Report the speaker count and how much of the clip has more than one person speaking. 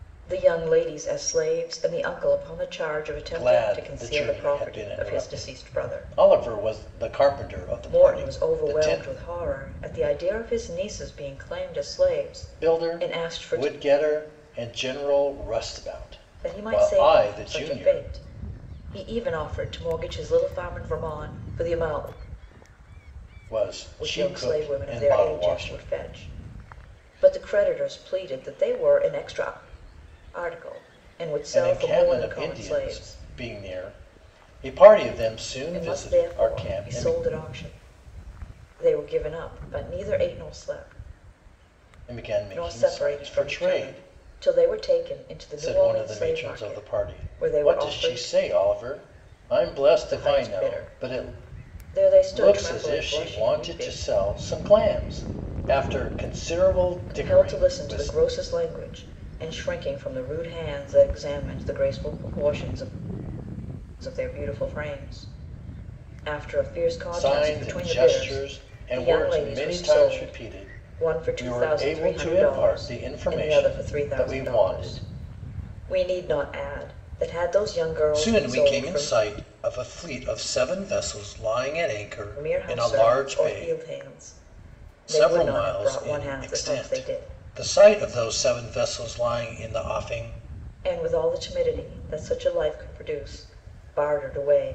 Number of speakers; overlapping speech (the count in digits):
2, about 34%